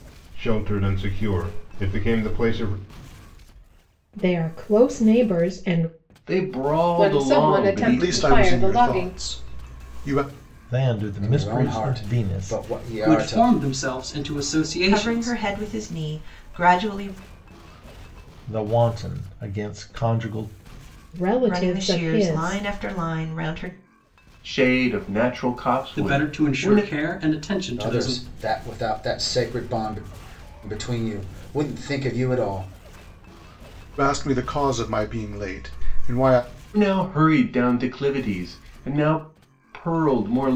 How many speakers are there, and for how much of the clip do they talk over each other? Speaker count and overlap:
nine, about 18%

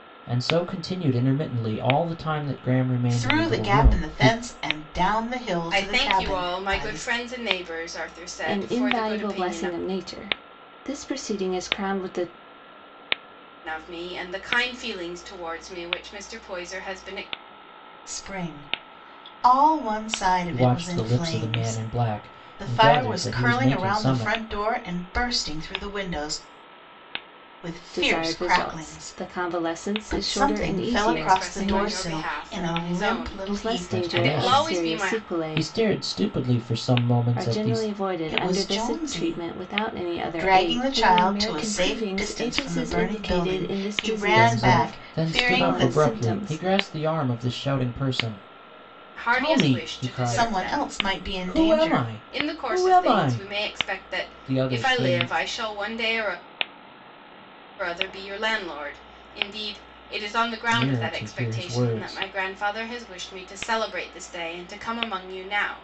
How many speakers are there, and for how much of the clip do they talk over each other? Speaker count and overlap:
four, about 45%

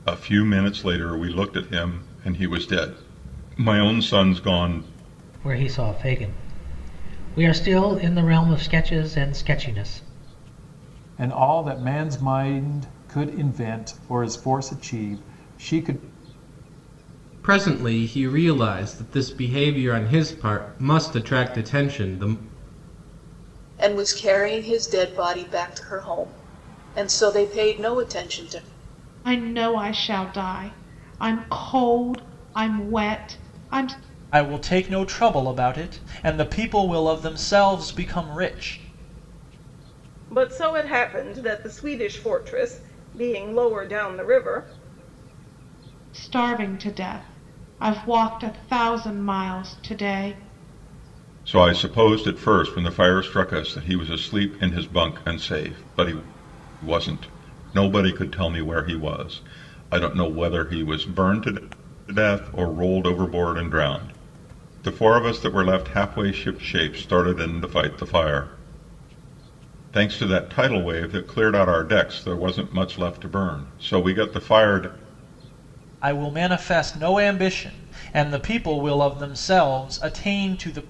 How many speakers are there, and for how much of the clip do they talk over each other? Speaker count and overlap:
eight, no overlap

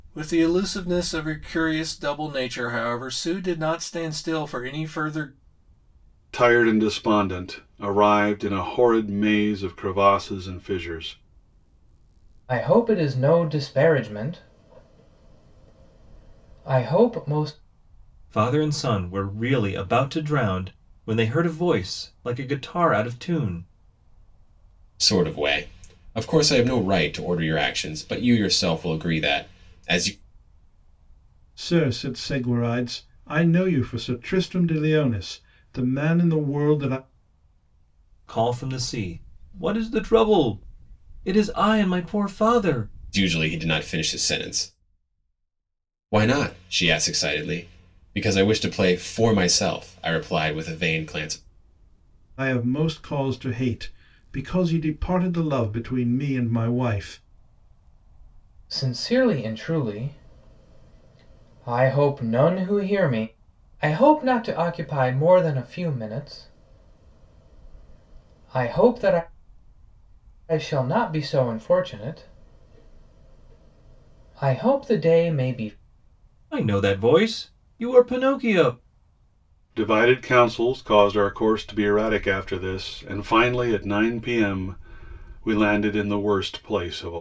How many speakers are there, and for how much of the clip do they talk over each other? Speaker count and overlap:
six, no overlap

